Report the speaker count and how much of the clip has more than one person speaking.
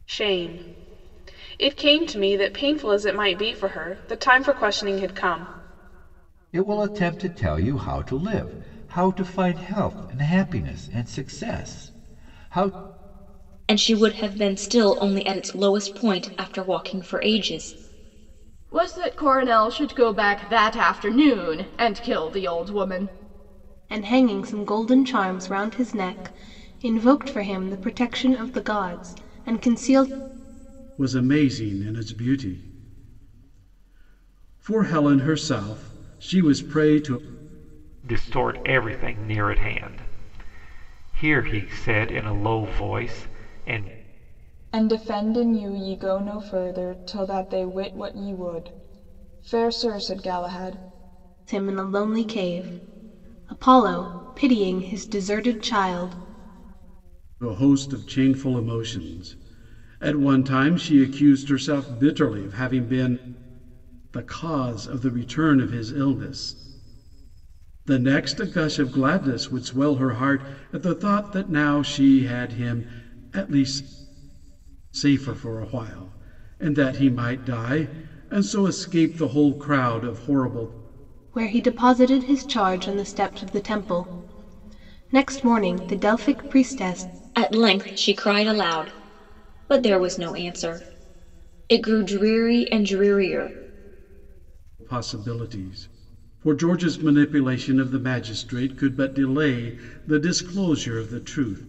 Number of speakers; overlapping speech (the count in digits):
8, no overlap